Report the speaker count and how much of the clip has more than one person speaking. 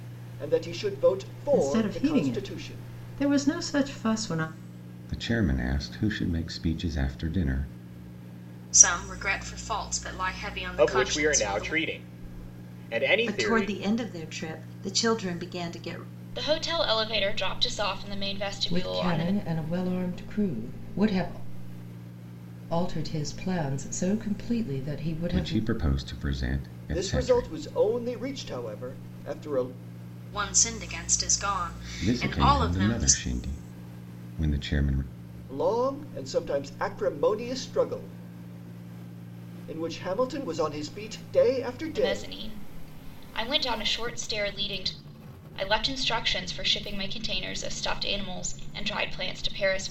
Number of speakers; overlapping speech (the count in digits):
8, about 12%